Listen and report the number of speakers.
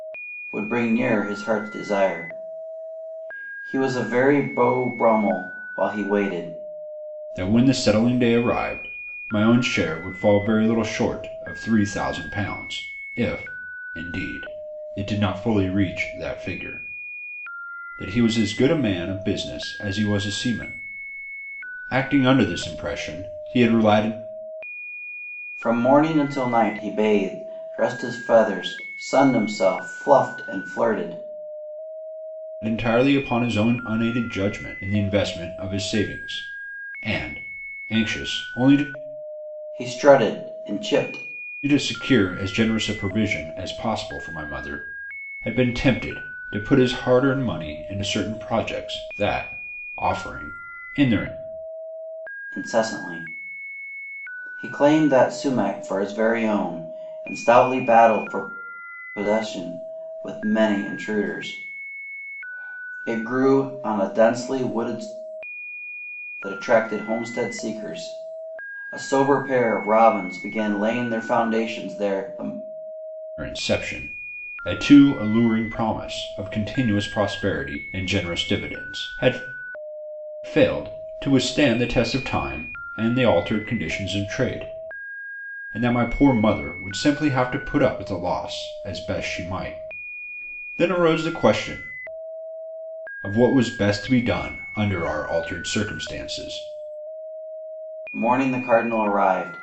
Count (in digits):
2